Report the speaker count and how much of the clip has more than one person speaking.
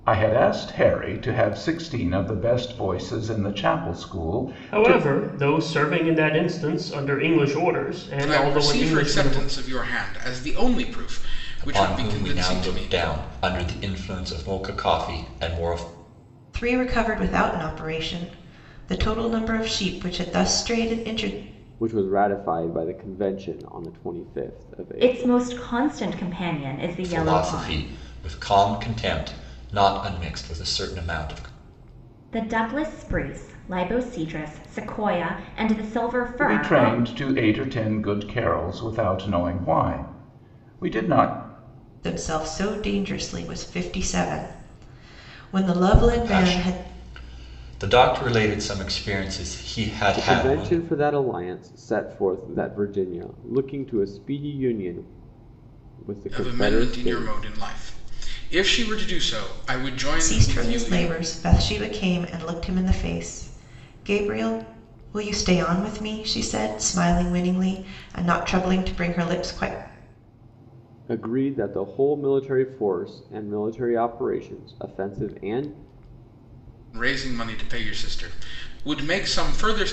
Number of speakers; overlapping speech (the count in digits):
7, about 11%